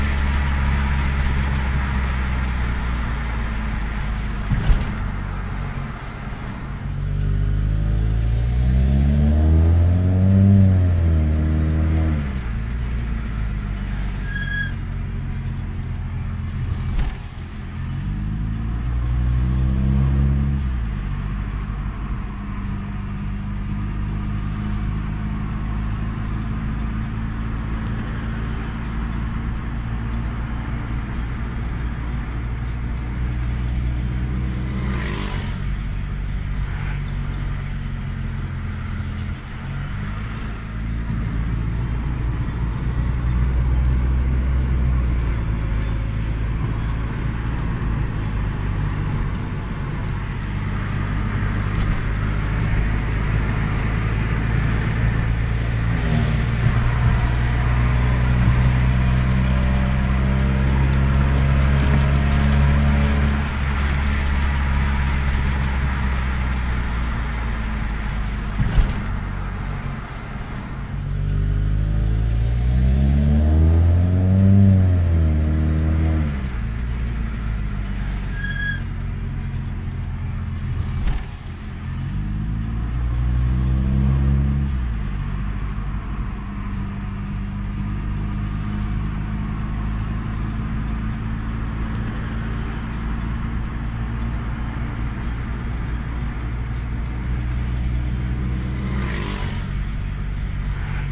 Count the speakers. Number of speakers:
zero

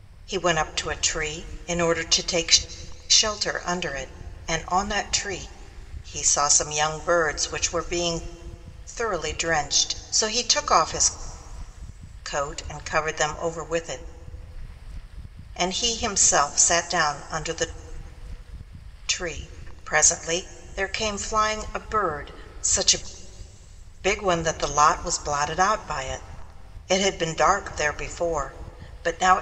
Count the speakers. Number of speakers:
one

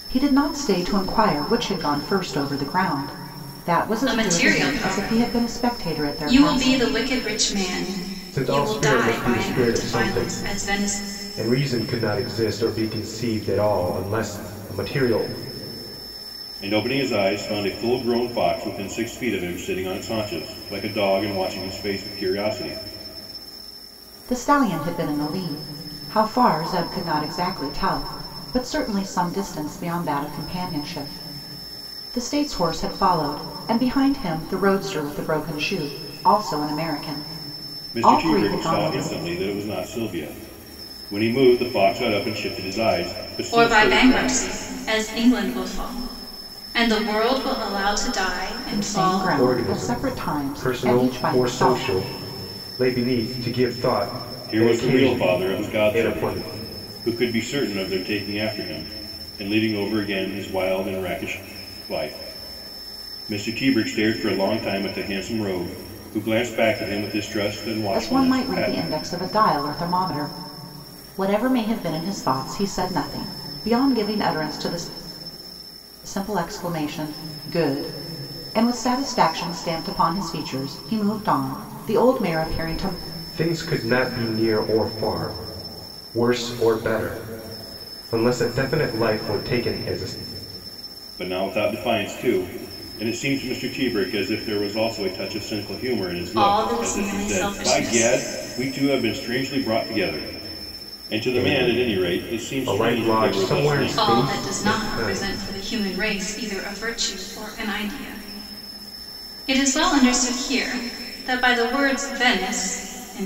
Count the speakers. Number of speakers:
four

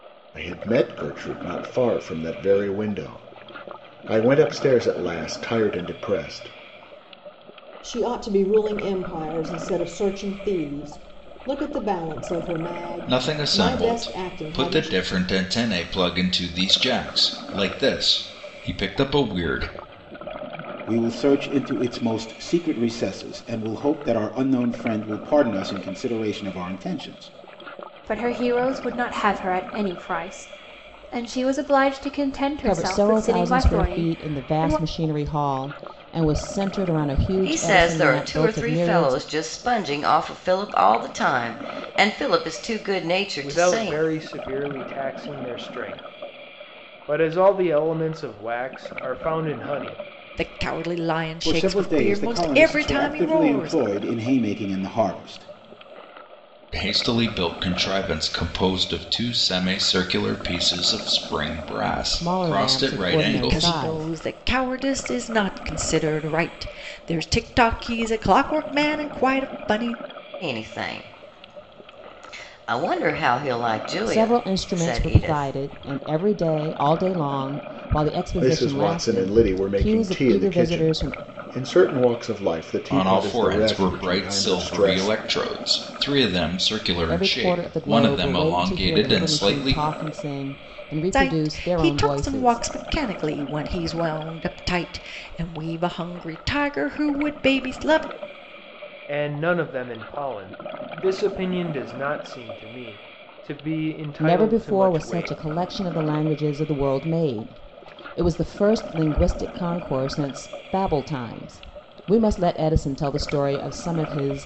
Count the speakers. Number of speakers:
nine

